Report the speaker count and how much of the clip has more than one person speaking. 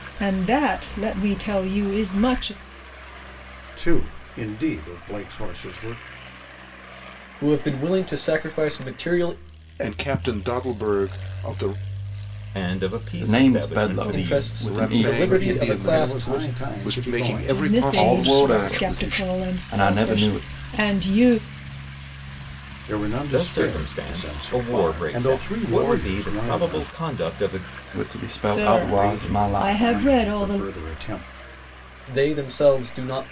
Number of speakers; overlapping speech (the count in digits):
6, about 40%